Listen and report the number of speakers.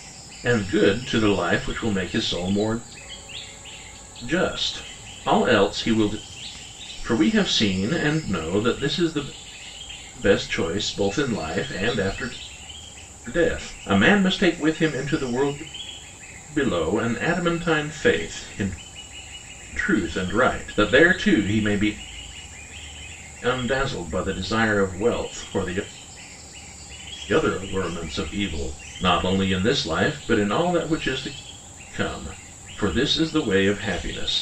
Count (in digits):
1